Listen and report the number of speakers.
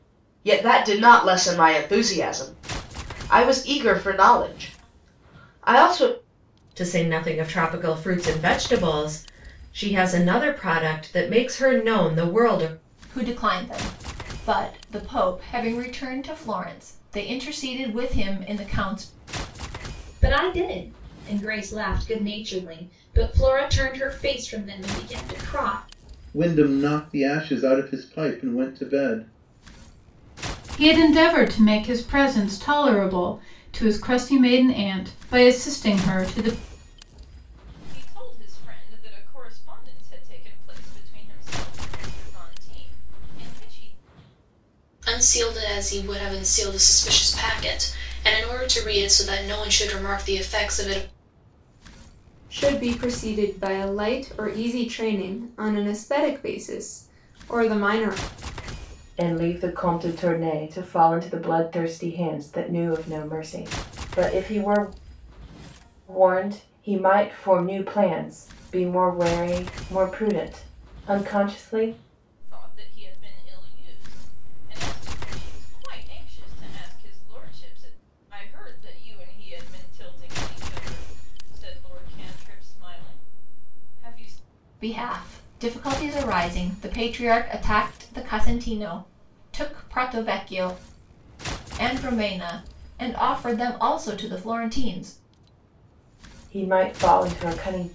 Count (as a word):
ten